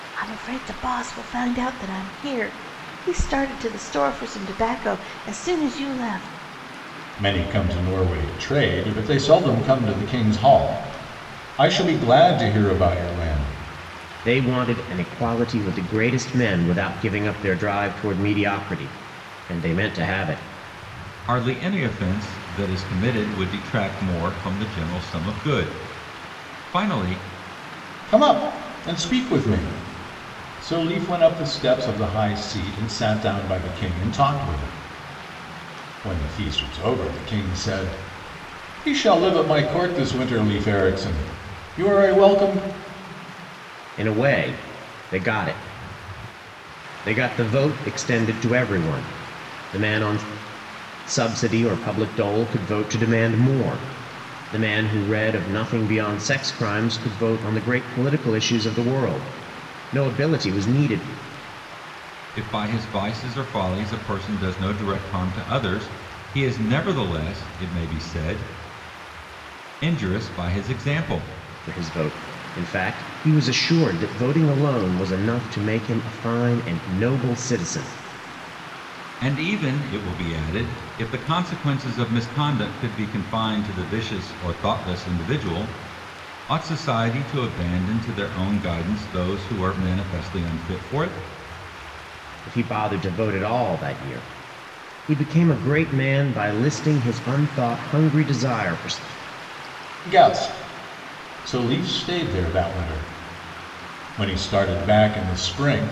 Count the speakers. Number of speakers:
4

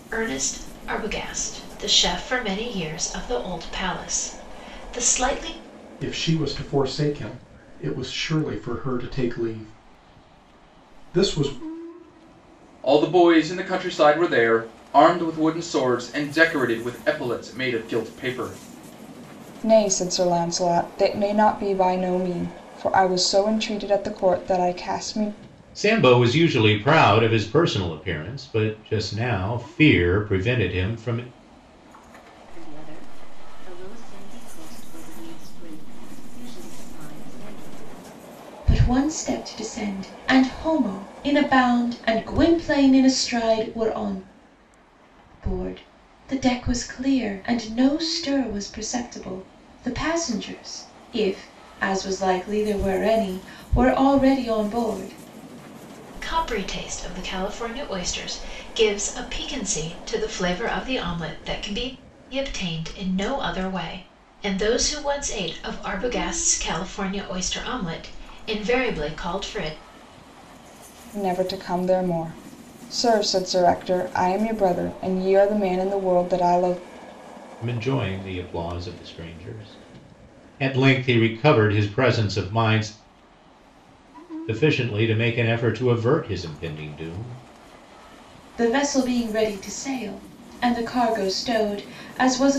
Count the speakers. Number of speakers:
7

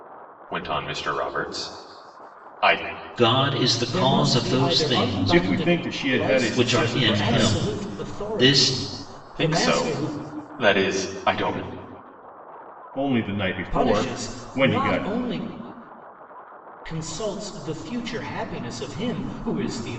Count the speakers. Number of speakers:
4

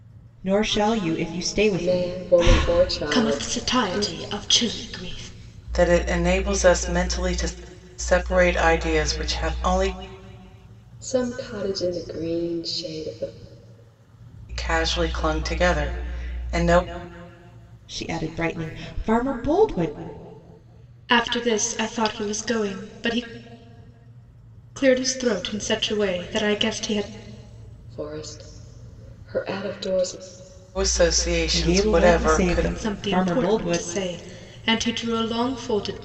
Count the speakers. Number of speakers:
4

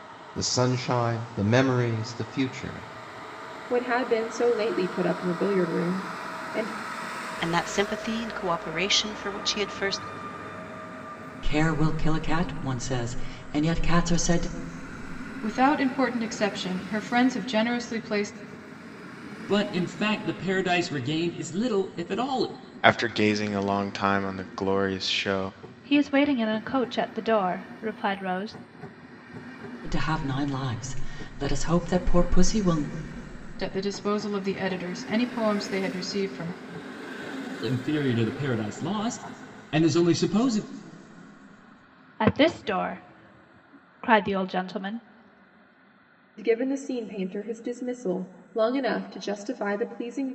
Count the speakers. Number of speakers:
8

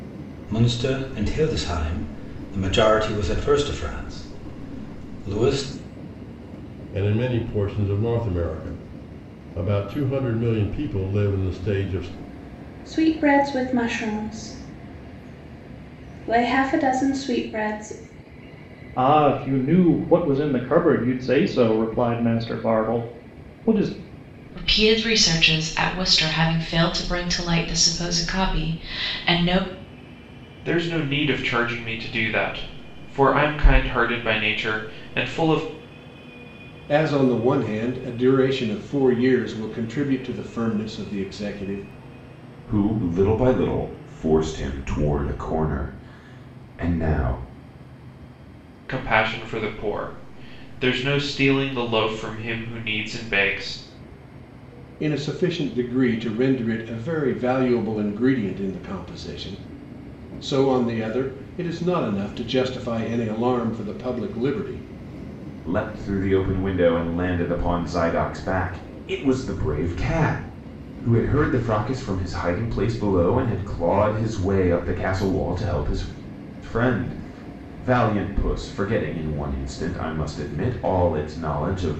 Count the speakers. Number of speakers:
8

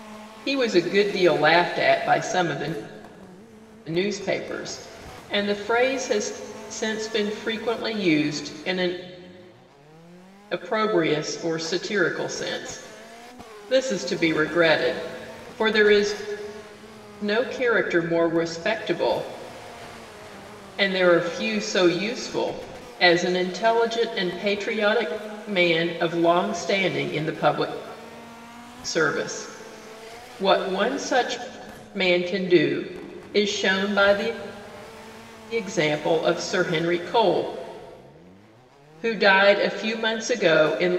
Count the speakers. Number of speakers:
1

